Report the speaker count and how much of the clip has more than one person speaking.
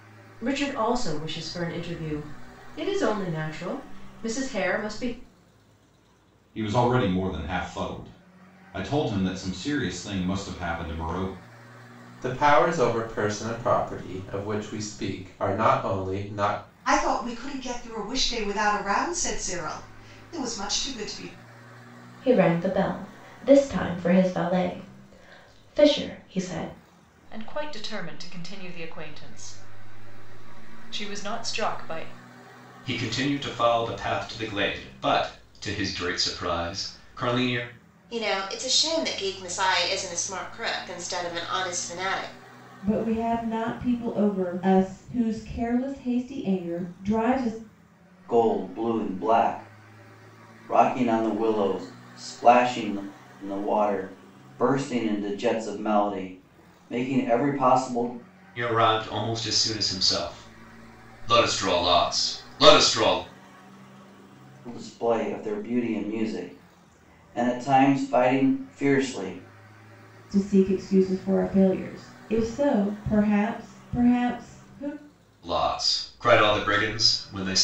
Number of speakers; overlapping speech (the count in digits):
10, no overlap